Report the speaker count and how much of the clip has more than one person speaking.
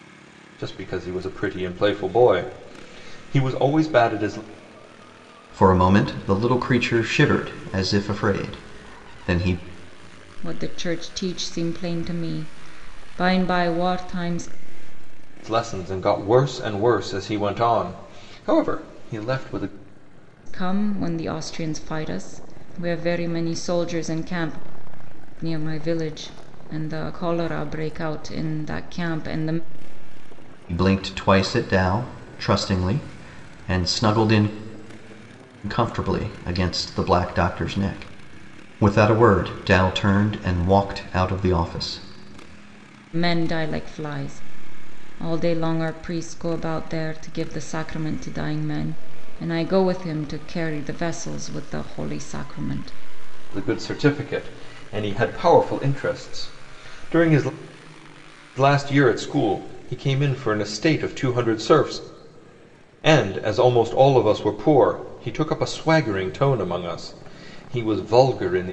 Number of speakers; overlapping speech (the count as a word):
three, no overlap